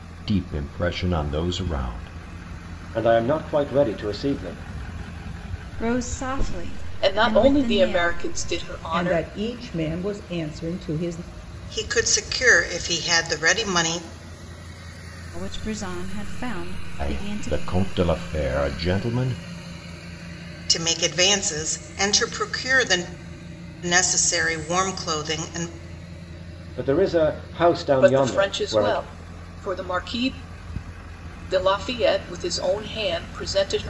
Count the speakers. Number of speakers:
6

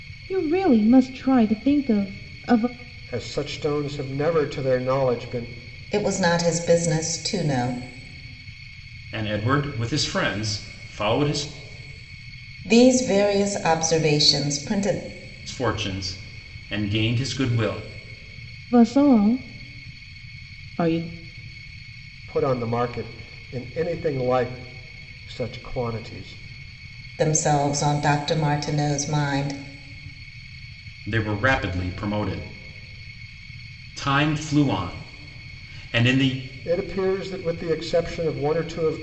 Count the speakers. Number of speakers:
4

